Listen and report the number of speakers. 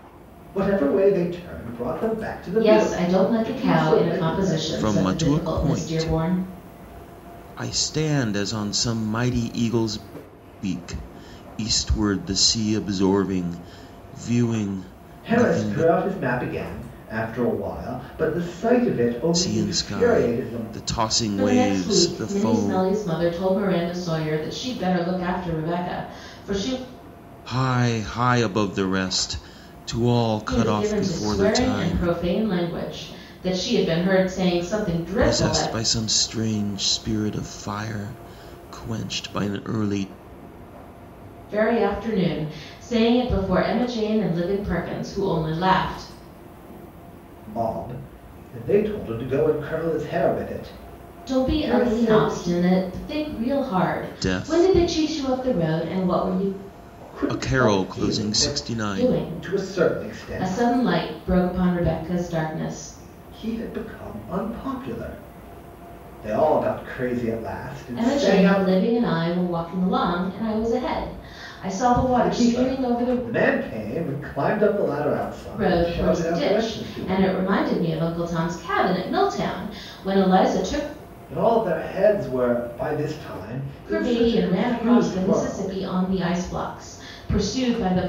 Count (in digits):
3